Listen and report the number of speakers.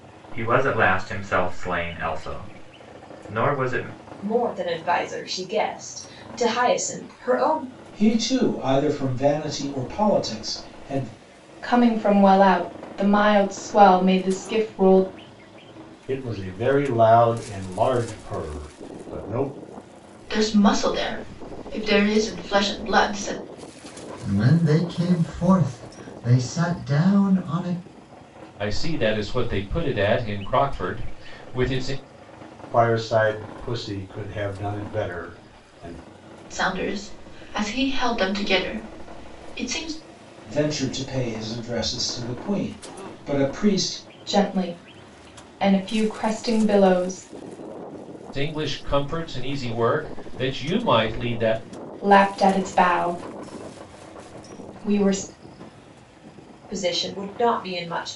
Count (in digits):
8